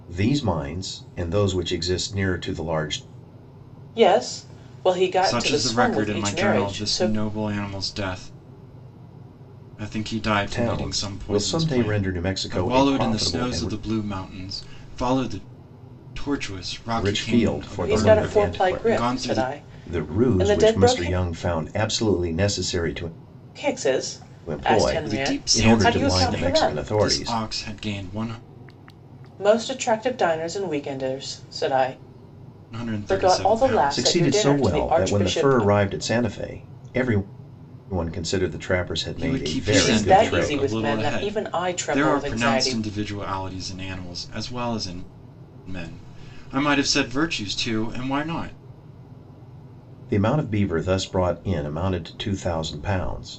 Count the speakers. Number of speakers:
three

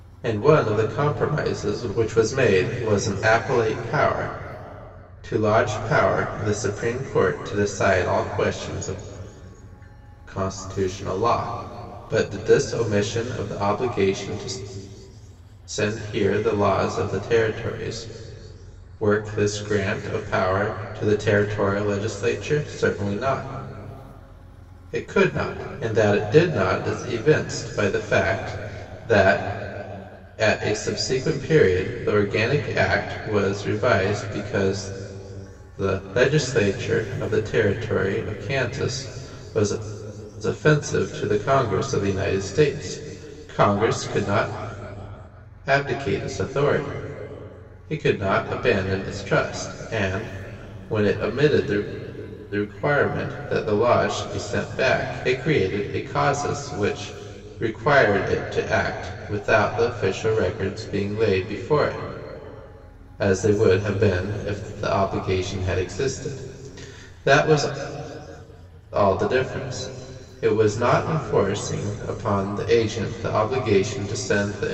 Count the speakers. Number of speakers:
one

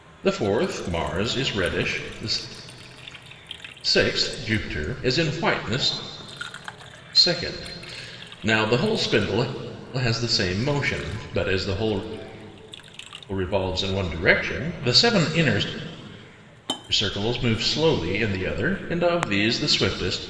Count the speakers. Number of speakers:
one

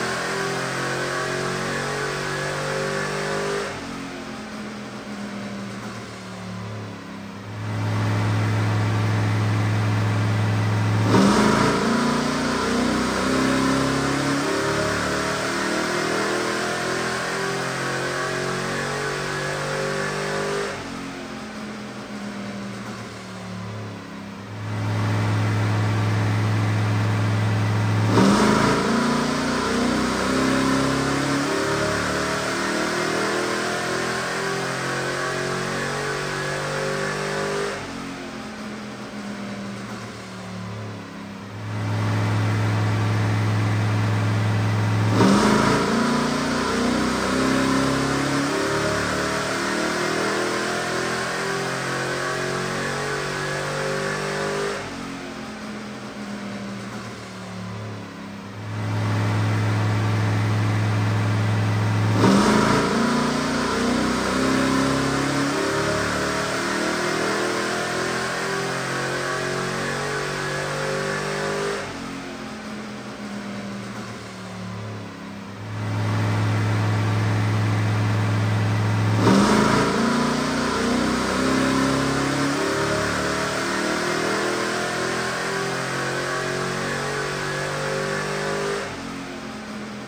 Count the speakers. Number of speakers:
zero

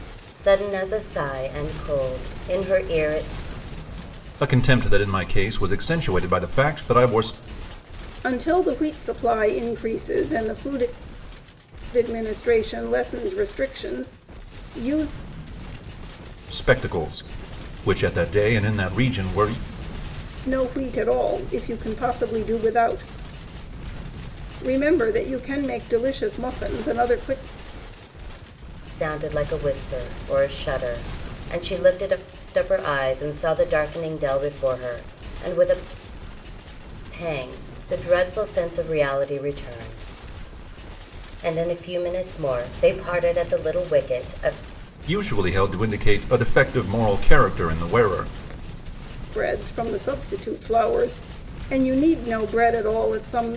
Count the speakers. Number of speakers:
three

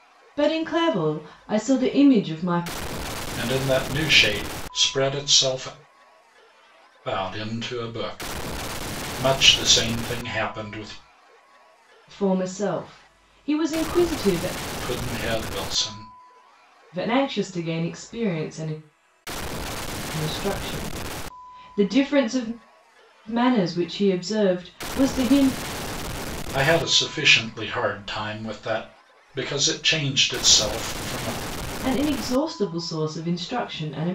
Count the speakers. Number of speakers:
two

